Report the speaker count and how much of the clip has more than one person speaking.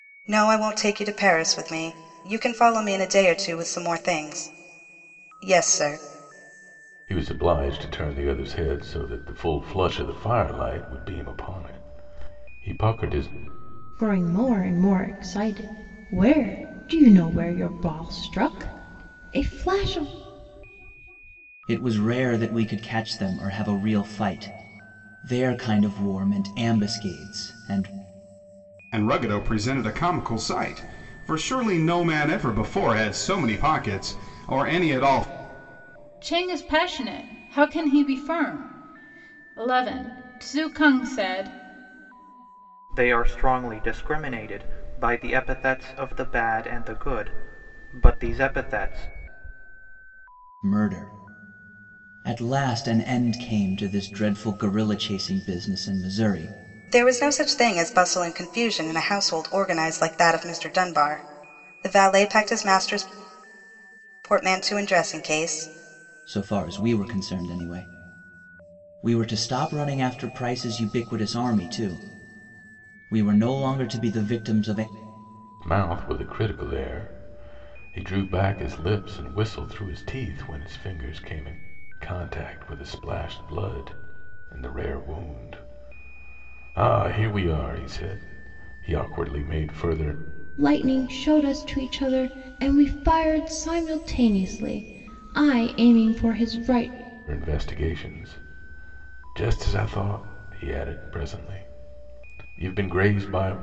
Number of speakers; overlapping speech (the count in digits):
7, no overlap